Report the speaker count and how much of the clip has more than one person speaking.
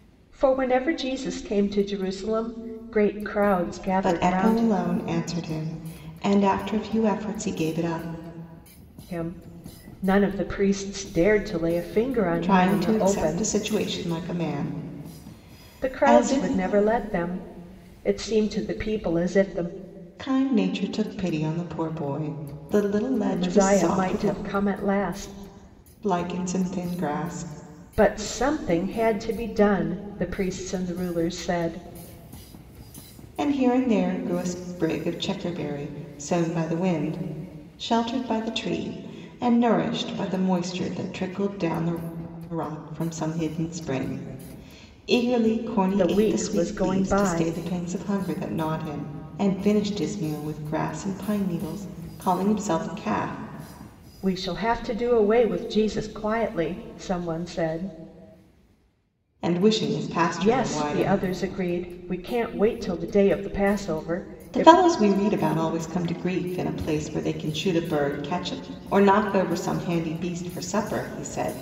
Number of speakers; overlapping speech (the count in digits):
2, about 9%